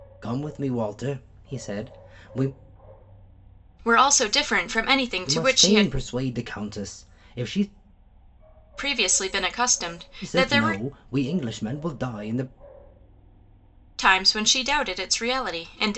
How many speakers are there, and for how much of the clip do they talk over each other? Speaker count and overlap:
2, about 8%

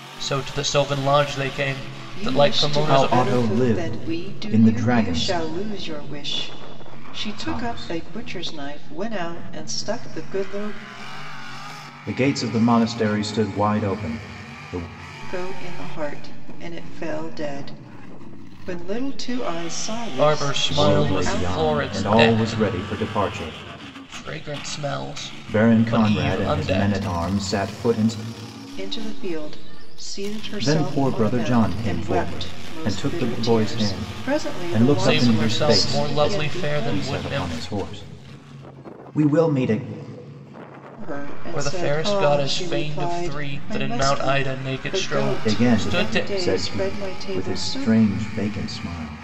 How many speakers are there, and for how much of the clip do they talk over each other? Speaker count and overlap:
3, about 43%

